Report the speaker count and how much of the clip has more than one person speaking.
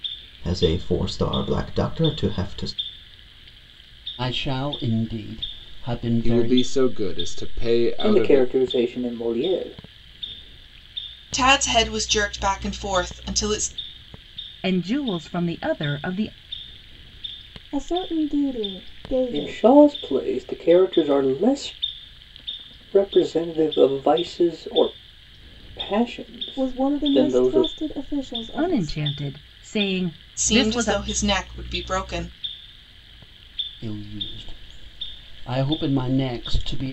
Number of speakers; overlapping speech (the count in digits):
7, about 10%